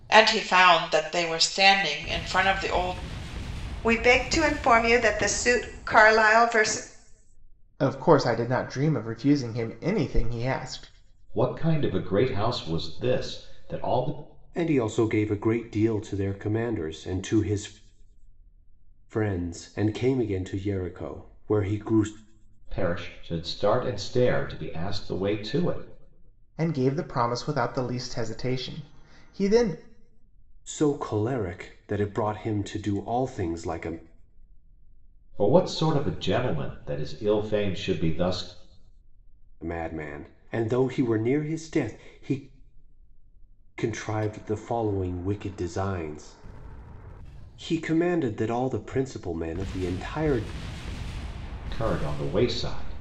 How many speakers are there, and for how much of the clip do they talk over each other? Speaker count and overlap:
five, no overlap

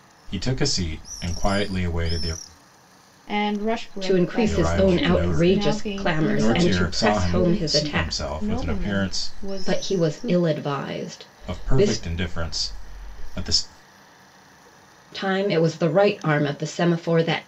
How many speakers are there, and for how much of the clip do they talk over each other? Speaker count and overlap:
three, about 38%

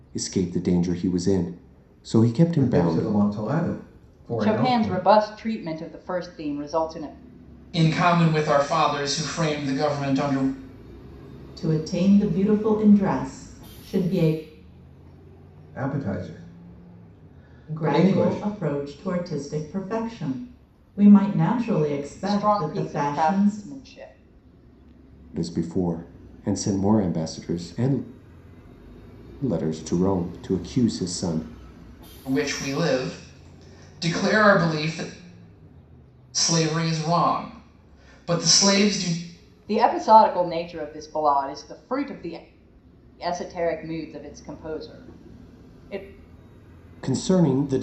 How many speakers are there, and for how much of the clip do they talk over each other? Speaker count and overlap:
five, about 7%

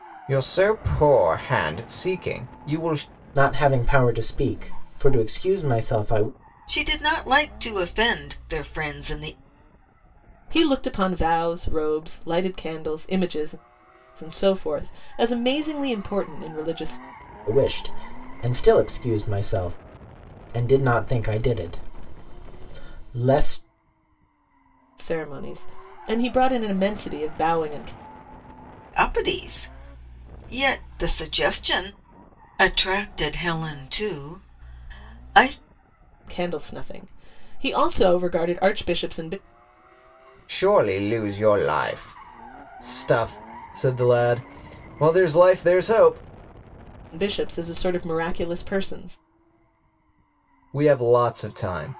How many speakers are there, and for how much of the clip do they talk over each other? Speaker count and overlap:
four, no overlap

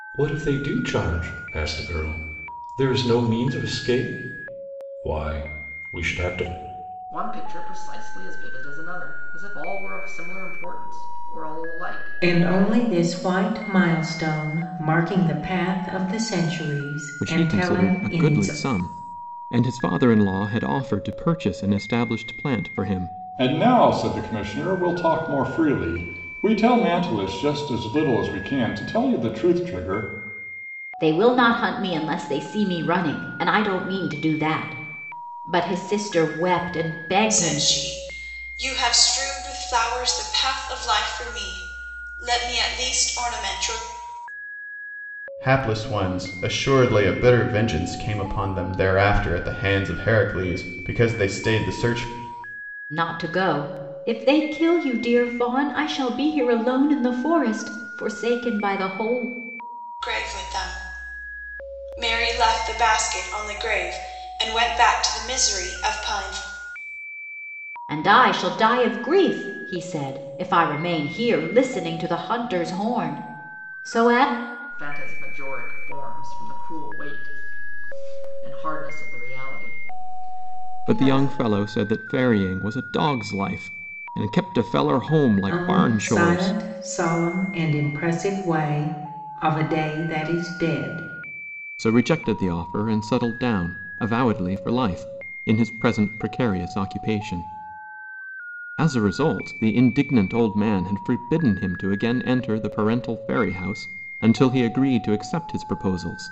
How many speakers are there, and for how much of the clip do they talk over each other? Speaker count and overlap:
eight, about 4%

